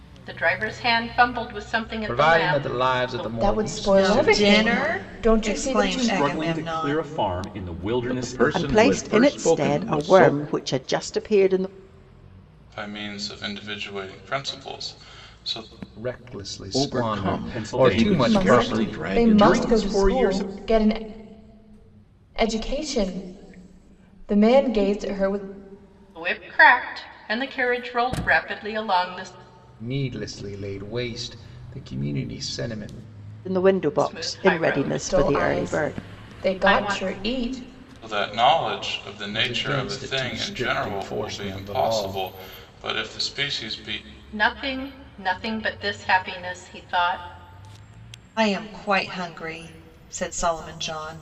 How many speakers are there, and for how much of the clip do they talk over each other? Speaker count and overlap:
8, about 34%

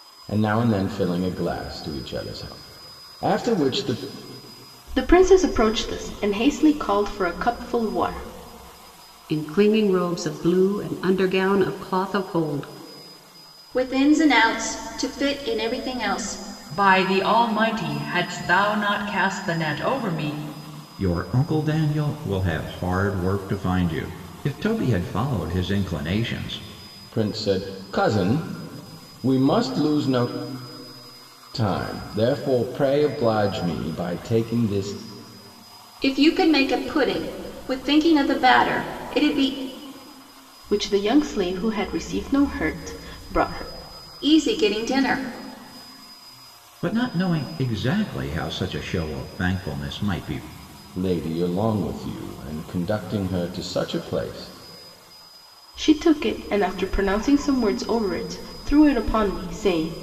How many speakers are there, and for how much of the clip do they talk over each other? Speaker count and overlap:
6, no overlap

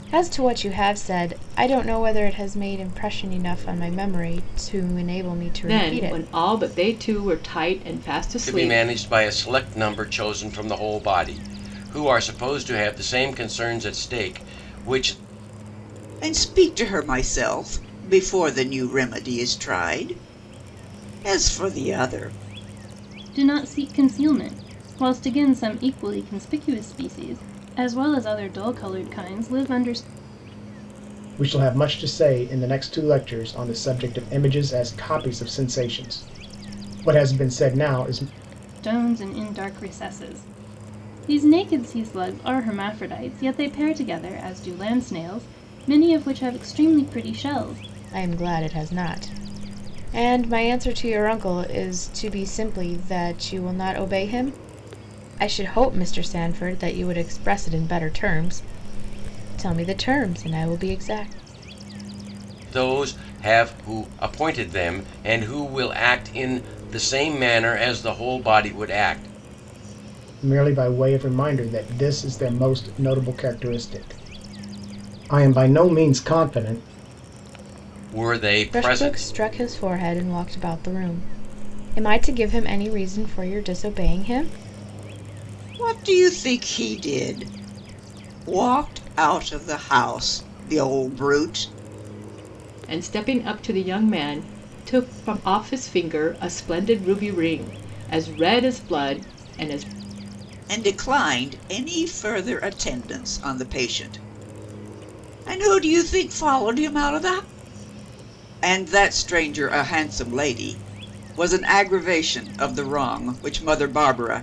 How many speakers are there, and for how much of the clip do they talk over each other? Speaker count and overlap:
6, about 2%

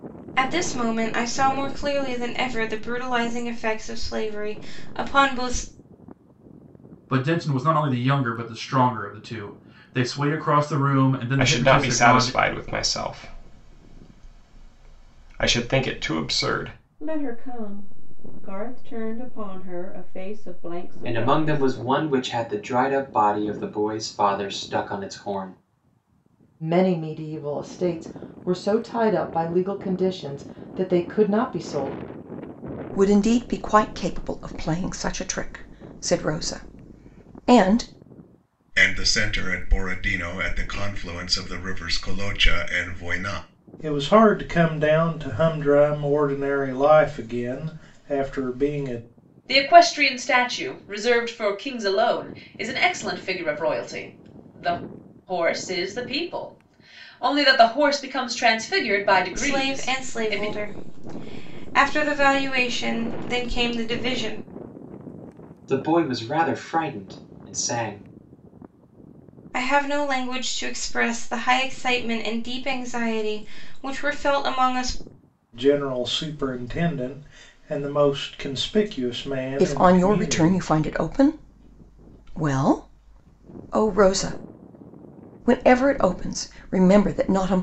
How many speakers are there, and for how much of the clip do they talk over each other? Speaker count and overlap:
10, about 4%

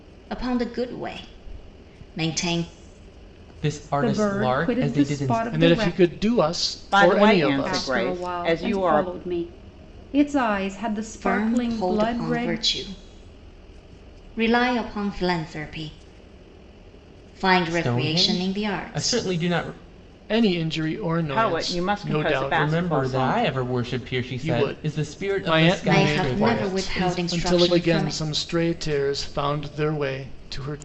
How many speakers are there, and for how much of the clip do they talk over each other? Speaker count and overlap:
5, about 42%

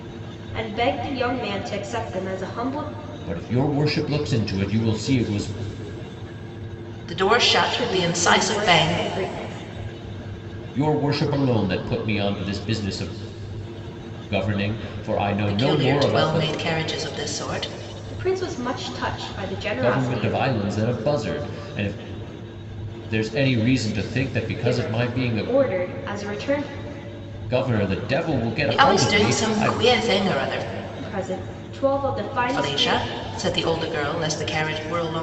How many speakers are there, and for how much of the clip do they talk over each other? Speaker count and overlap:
3, about 17%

